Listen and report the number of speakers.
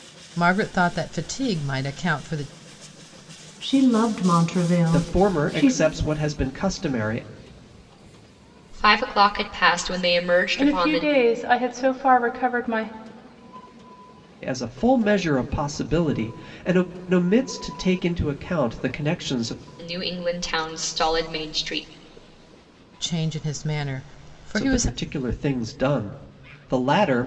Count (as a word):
five